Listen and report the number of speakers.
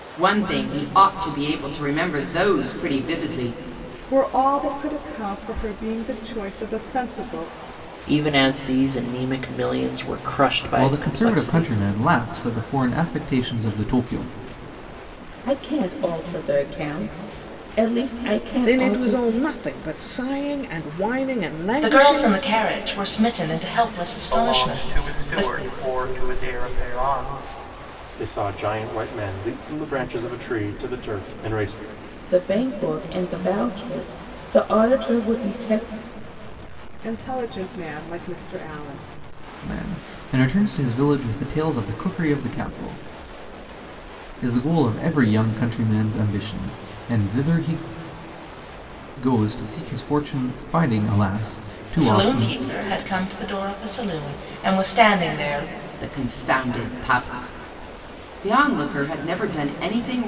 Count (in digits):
9